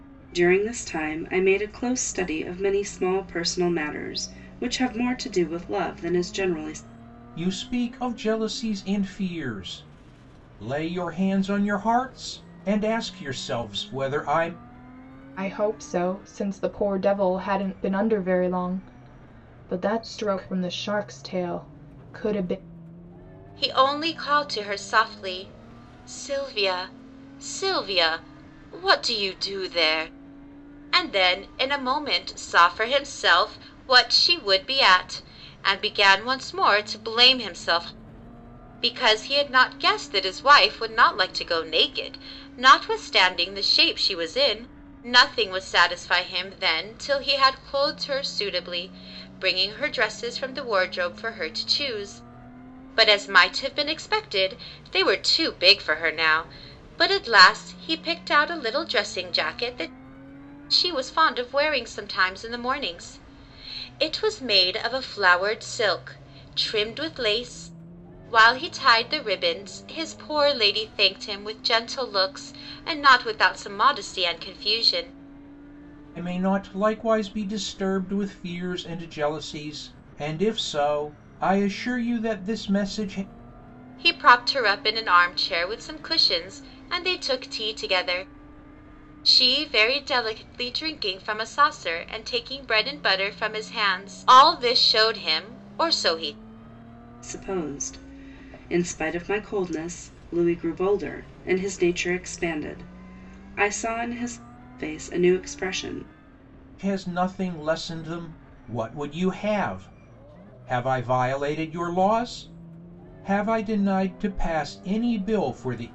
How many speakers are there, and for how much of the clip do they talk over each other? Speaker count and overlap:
four, no overlap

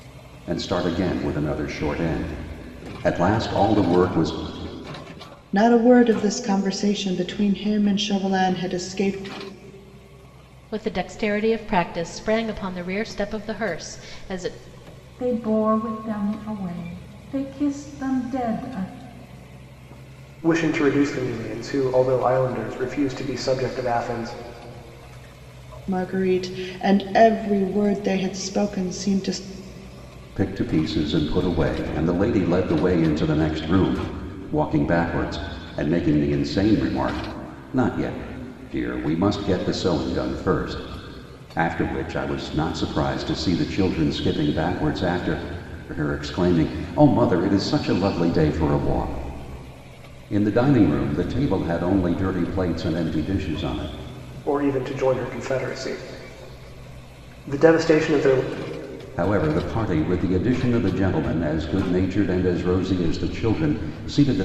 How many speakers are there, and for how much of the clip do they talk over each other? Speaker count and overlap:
five, no overlap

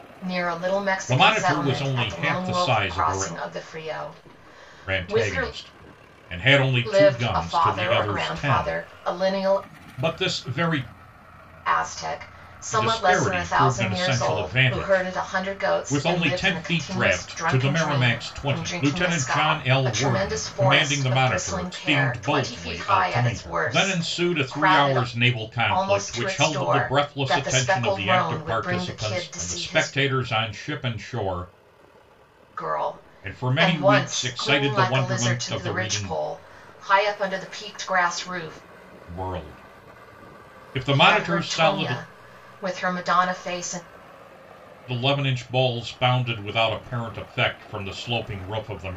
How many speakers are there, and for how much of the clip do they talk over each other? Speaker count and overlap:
two, about 52%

